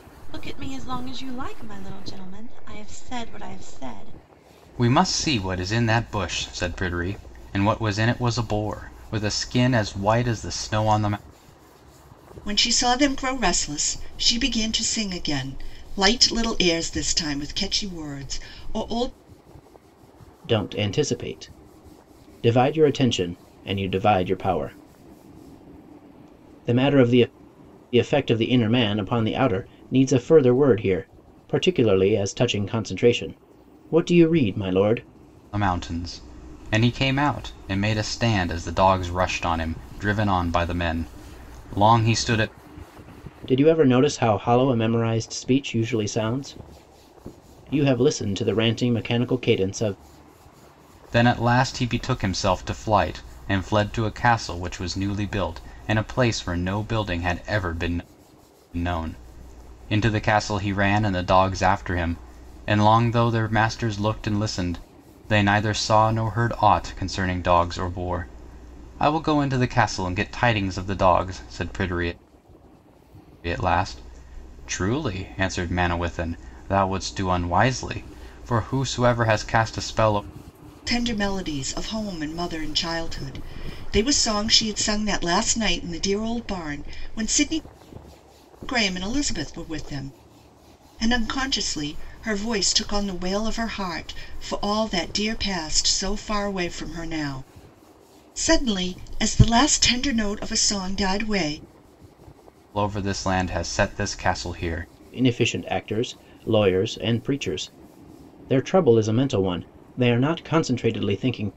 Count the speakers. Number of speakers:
four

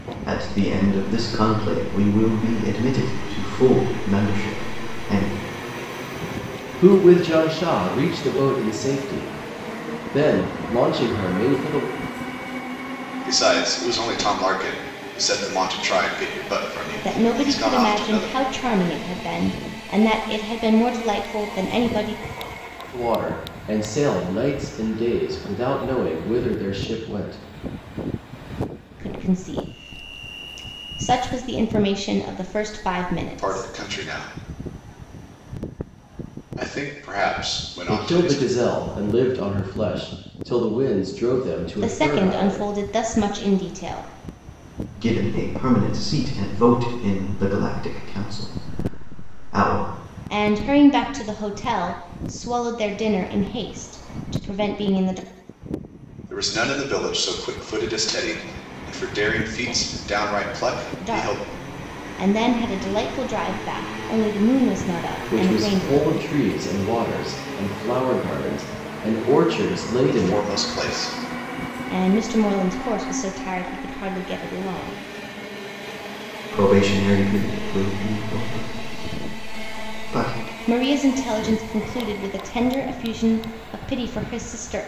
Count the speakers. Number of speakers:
four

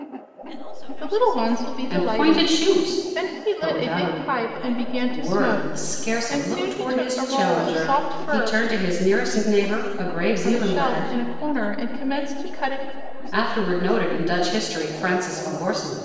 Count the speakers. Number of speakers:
three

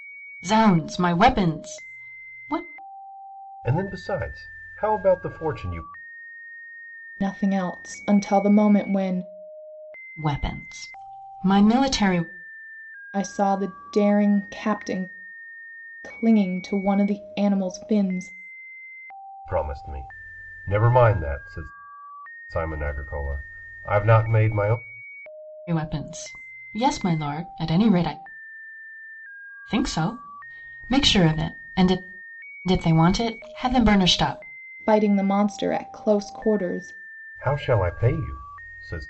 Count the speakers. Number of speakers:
three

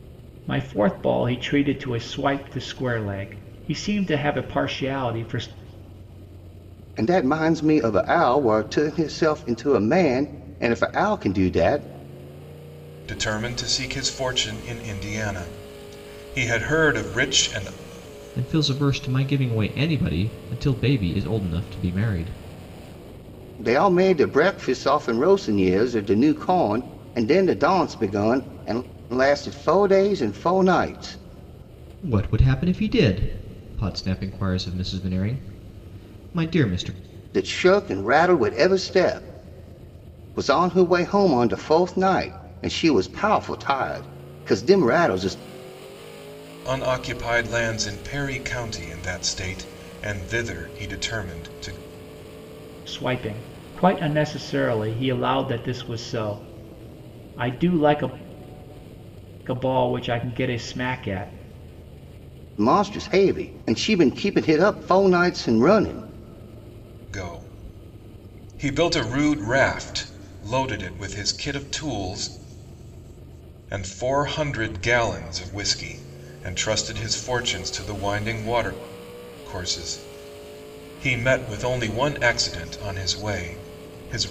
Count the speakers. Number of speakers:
four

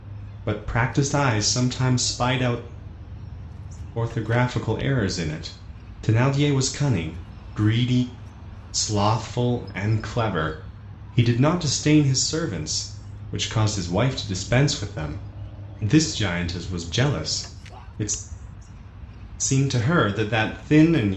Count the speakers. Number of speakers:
one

